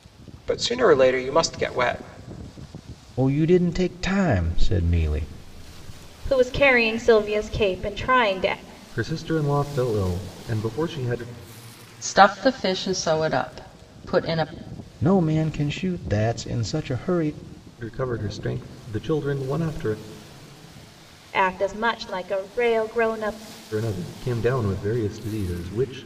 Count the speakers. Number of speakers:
5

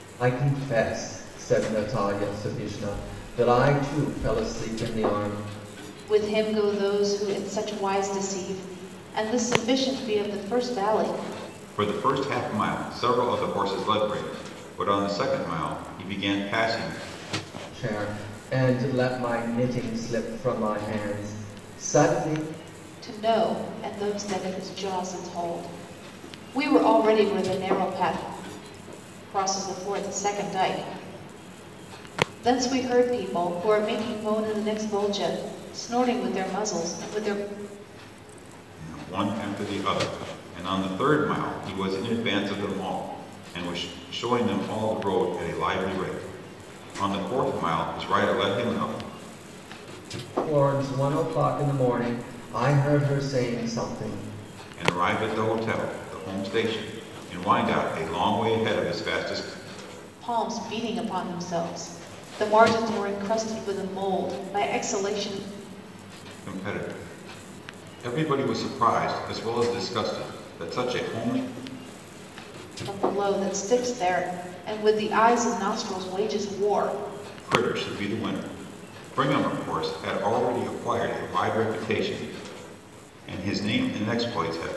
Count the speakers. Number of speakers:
3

